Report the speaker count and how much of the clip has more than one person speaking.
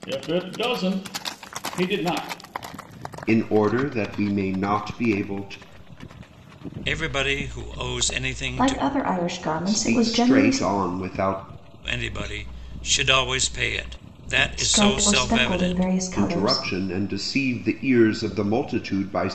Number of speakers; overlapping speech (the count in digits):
4, about 16%